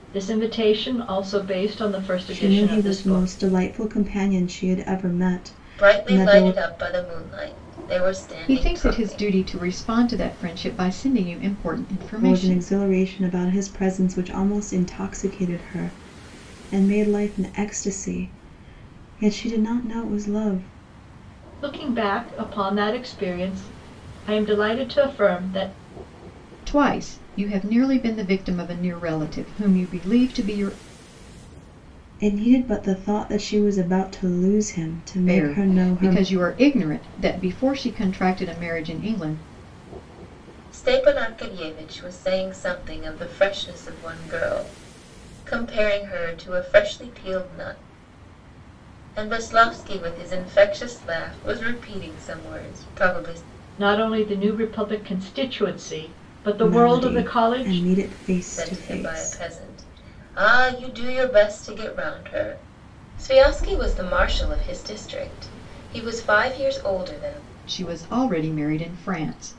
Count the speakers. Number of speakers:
four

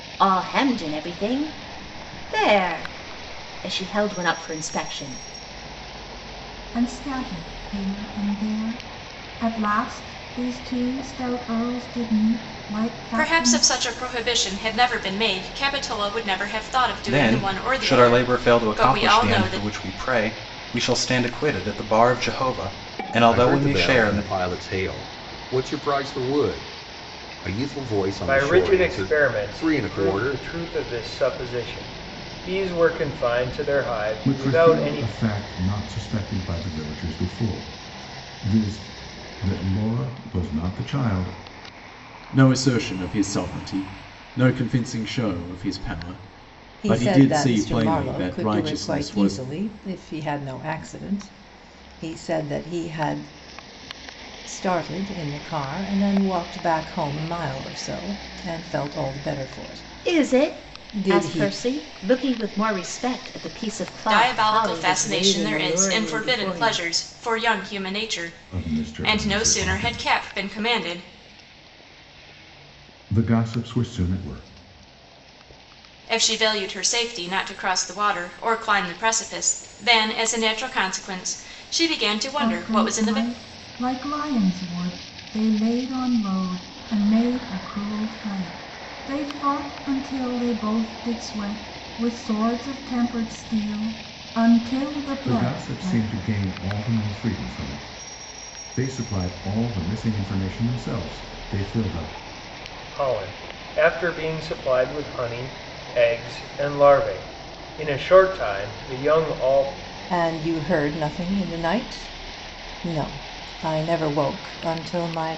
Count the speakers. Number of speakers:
nine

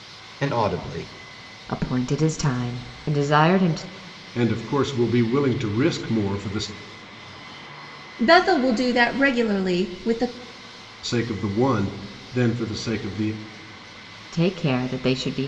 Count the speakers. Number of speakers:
four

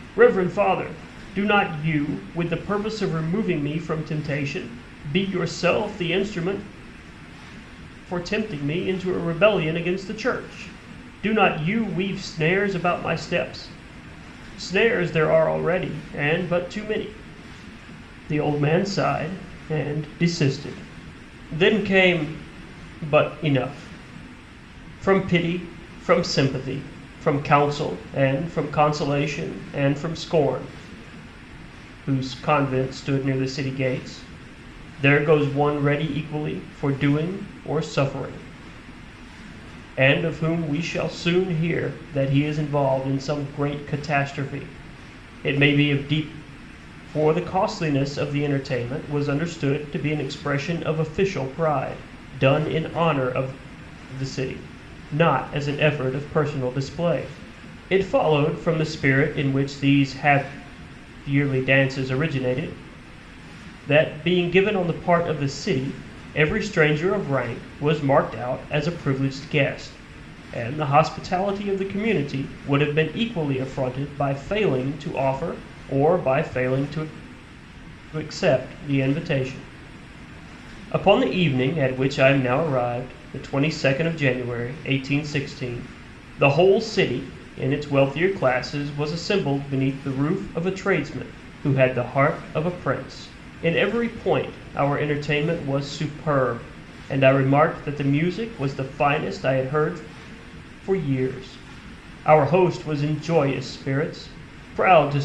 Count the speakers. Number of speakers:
one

